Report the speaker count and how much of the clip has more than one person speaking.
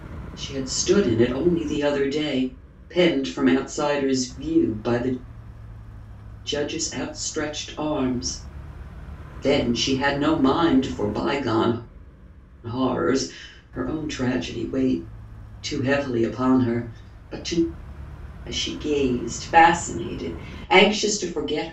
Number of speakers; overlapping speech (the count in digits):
1, no overlap